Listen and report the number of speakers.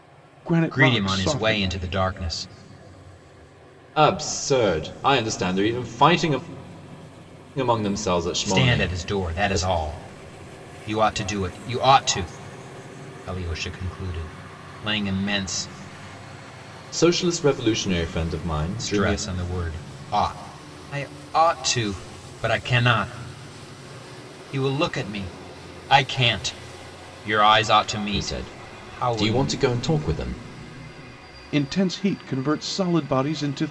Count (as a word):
three